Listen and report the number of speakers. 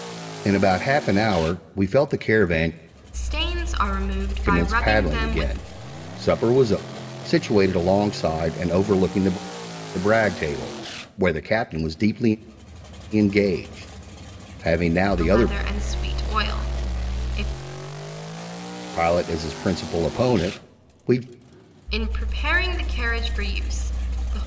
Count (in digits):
2